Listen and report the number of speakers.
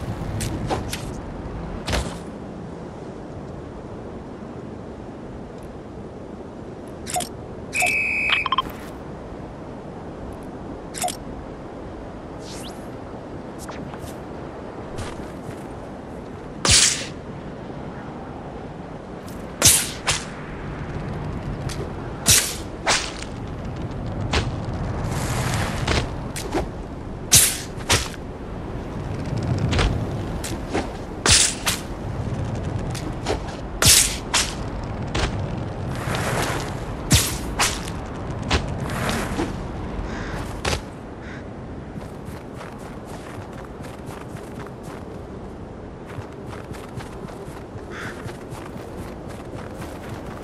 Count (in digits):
0